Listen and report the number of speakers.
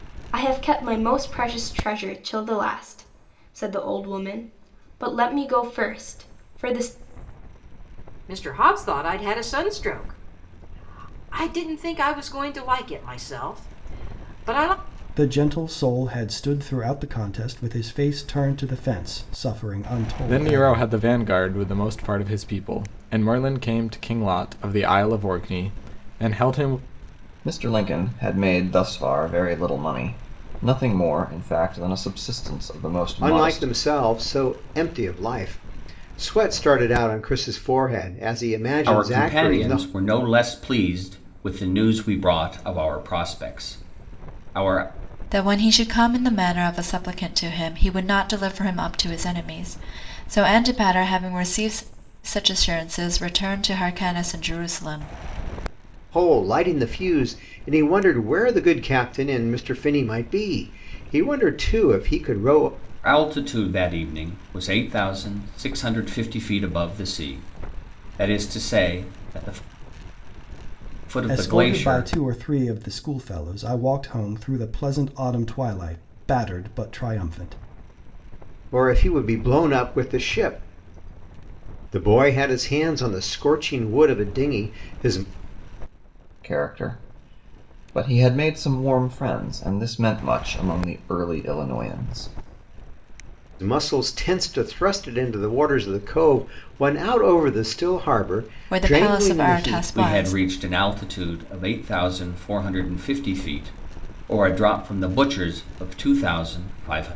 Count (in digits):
8